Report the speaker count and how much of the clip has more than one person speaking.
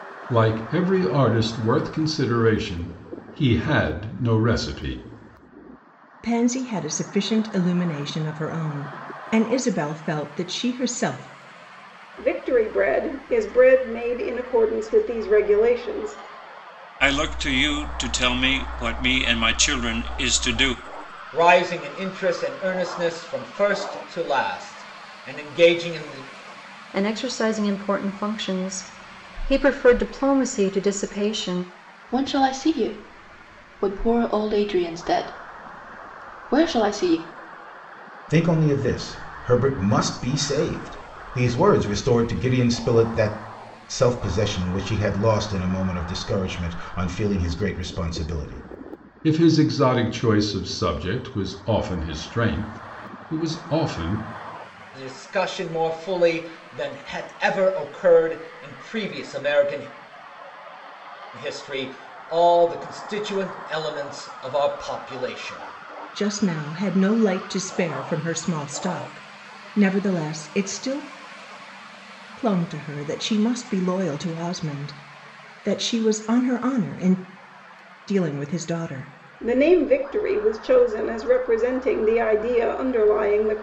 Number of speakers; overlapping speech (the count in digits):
8, no overlap